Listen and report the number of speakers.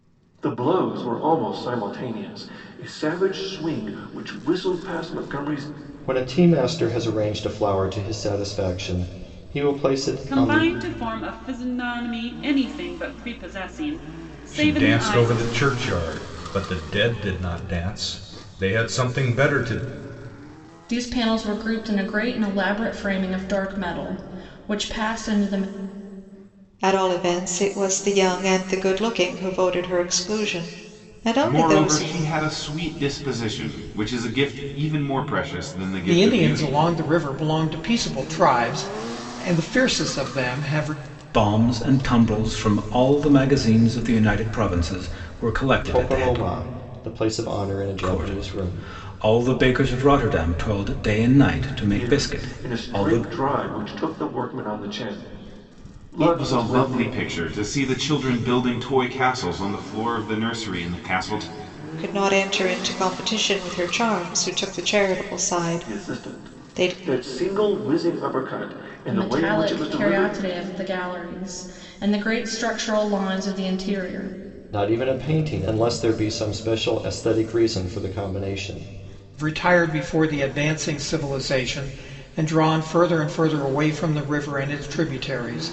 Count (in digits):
9